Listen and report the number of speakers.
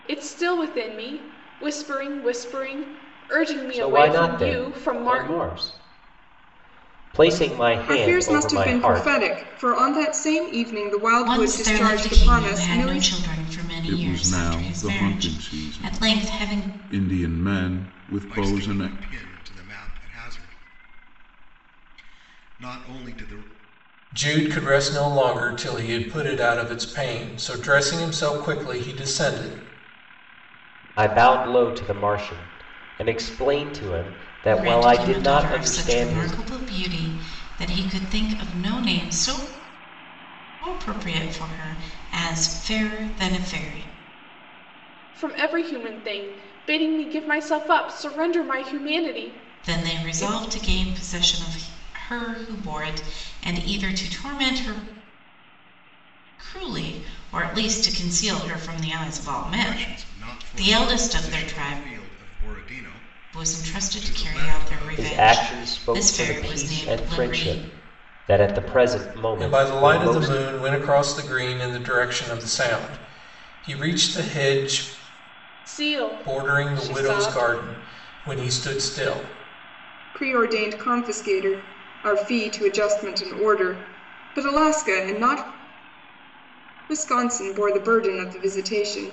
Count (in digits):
7